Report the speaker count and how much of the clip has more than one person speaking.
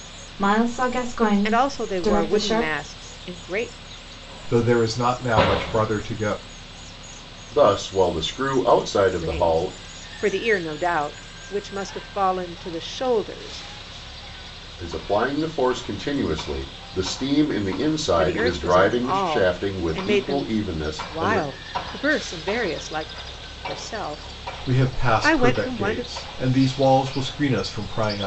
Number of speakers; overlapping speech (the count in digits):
4, about 22%